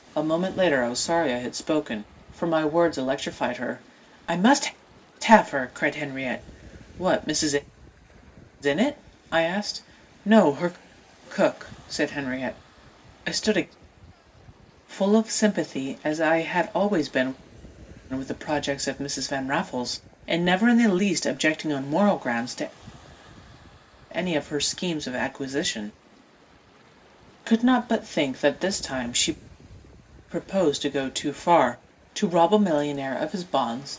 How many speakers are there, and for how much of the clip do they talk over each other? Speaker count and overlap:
one, no overlap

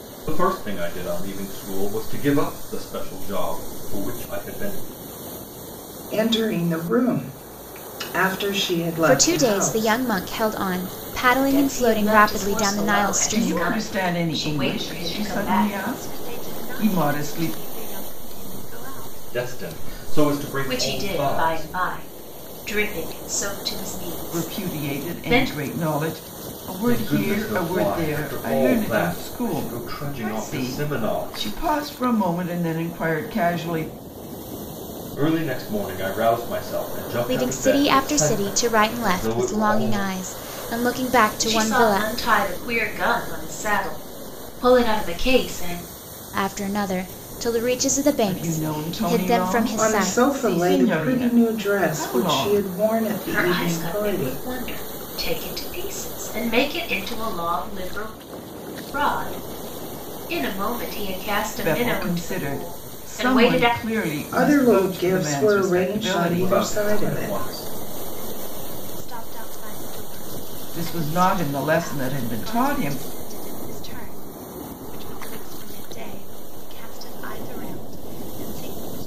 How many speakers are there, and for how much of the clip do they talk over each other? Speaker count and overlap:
six, about 41%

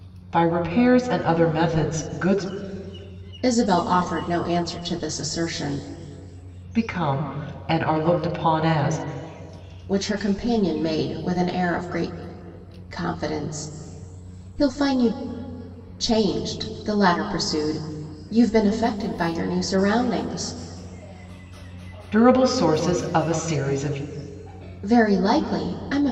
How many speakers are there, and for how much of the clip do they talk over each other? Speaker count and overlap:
two, no overlap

